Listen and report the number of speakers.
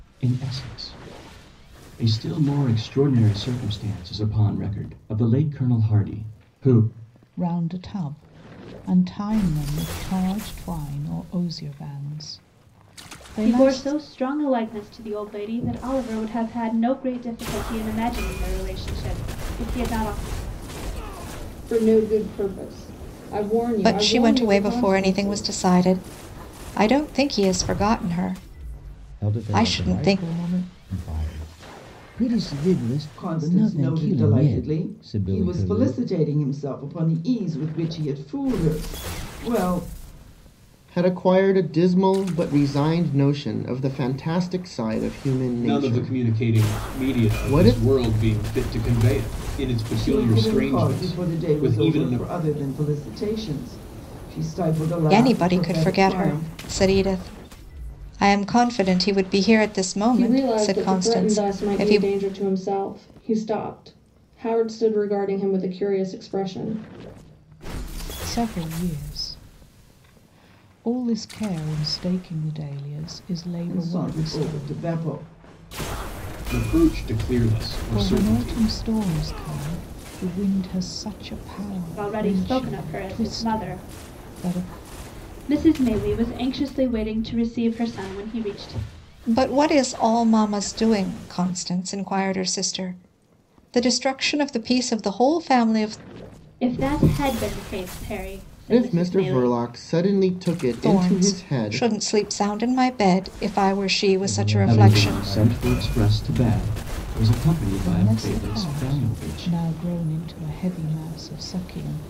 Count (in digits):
9